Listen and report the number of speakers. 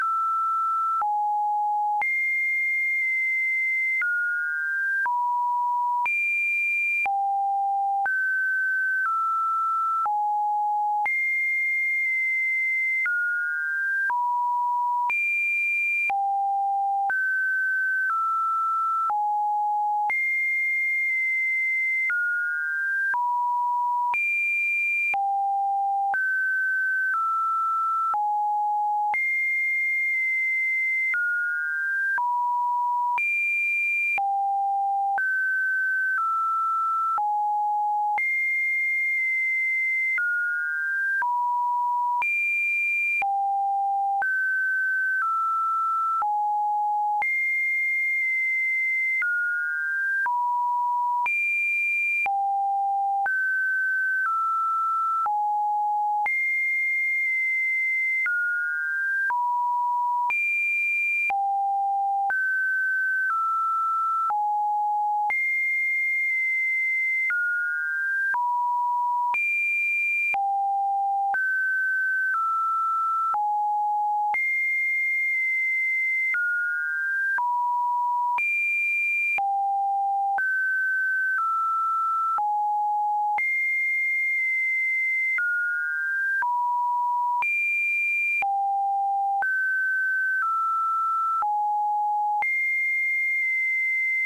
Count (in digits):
0